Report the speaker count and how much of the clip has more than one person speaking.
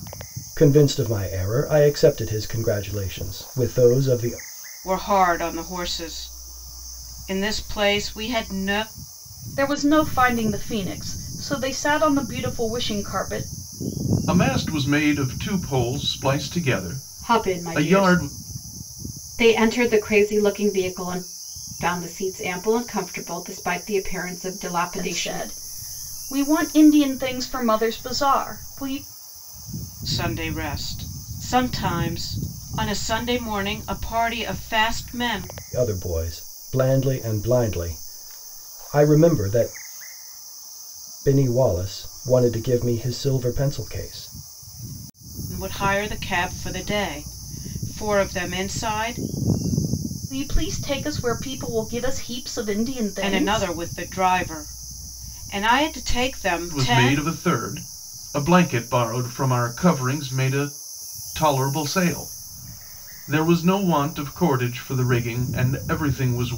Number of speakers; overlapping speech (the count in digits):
5, about 4%